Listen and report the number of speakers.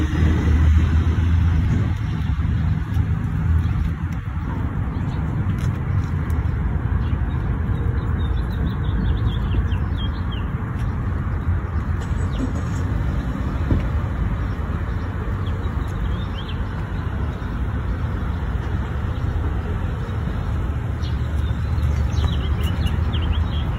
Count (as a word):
zero